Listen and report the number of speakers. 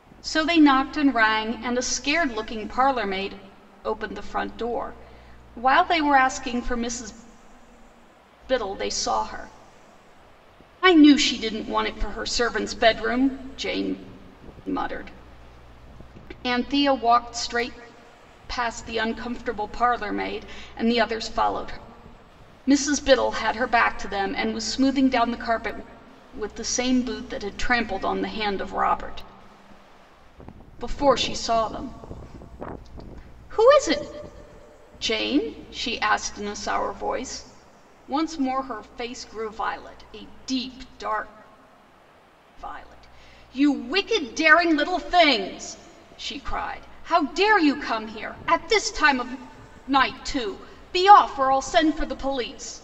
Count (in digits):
1